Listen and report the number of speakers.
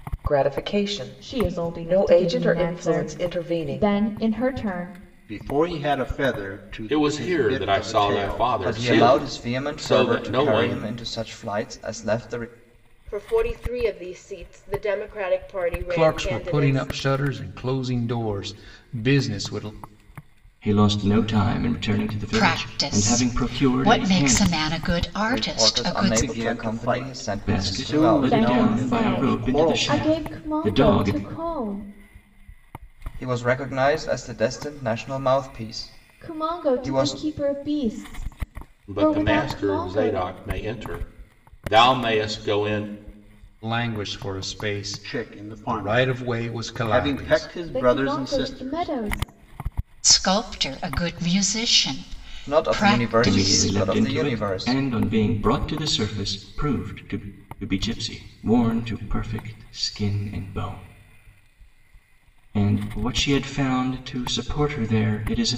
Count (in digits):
9